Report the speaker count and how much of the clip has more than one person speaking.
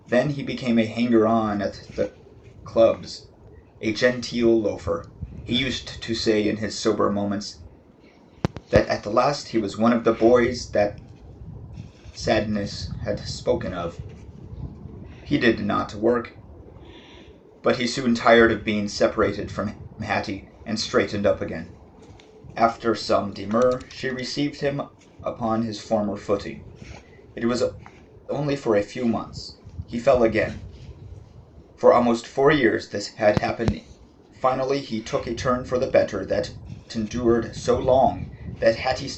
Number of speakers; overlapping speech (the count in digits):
1, no overlap